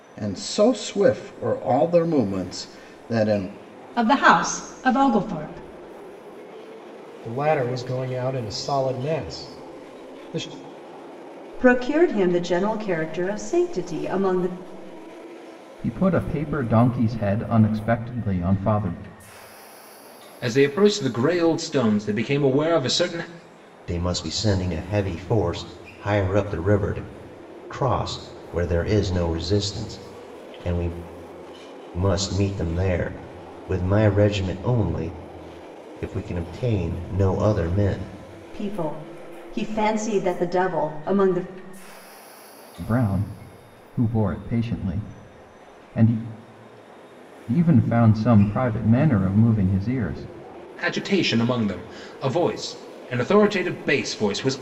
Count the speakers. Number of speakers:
7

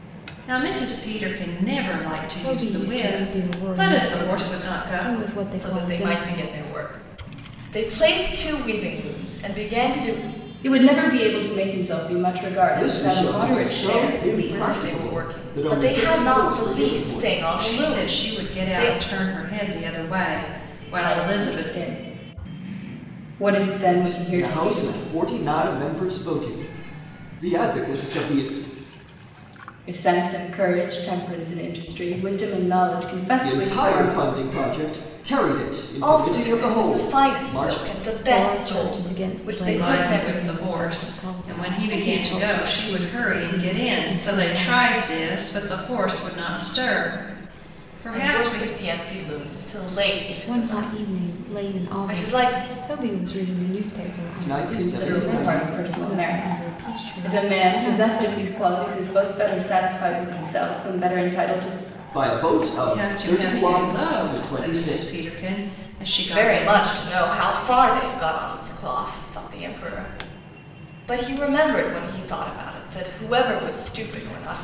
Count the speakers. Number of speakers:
5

